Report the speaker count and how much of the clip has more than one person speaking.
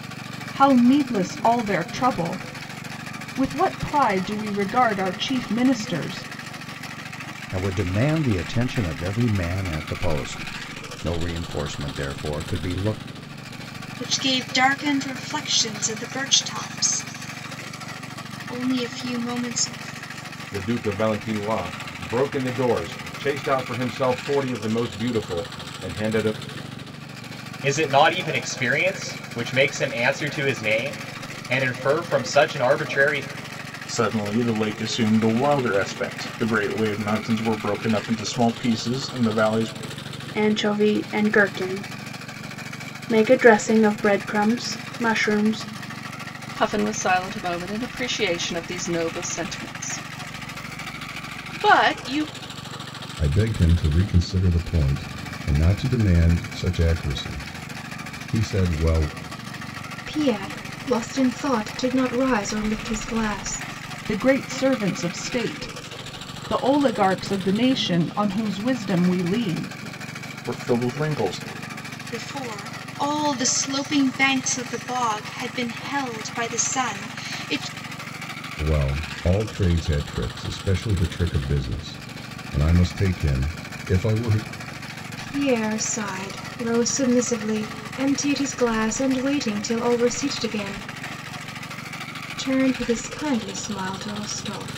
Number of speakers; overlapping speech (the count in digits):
10, no overlap